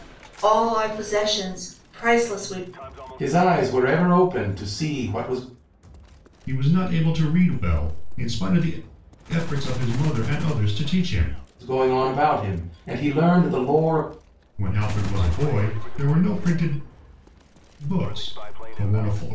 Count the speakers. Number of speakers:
three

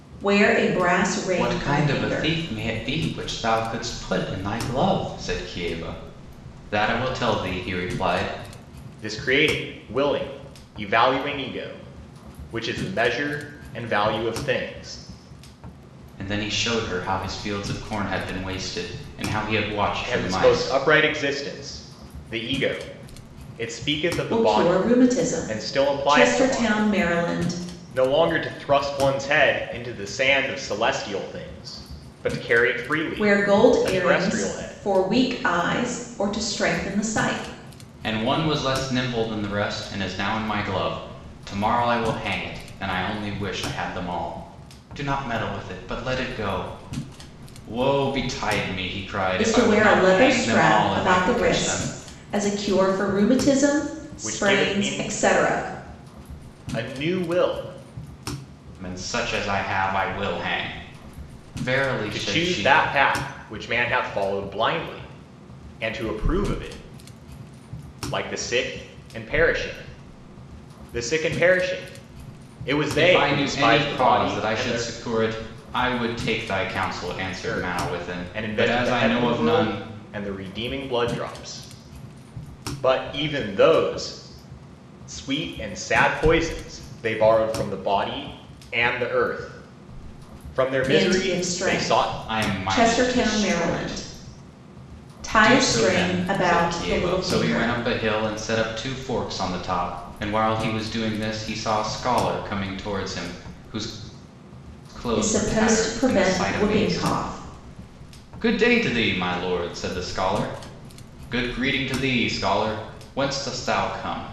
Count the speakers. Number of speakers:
three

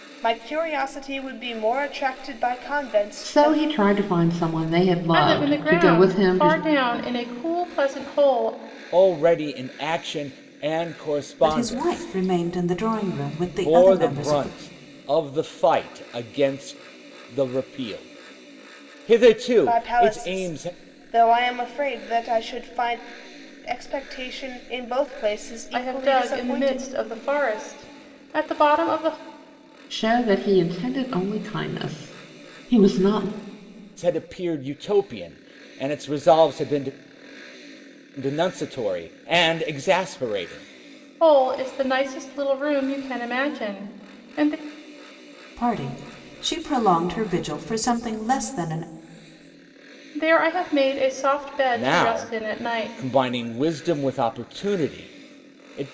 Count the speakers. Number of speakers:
five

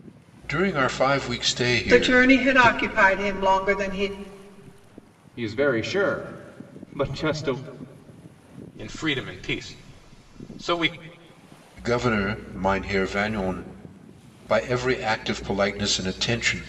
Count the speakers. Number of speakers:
four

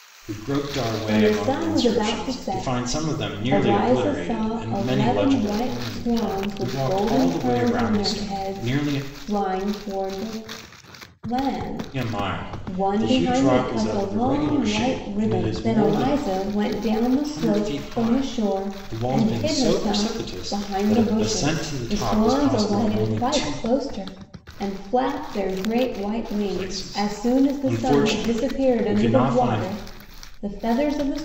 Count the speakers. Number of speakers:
two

